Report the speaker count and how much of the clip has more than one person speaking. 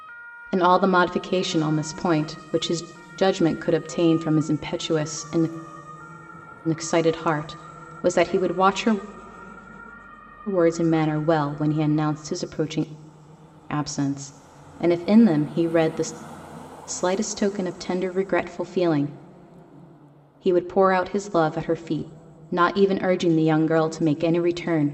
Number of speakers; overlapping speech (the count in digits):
1, no overlap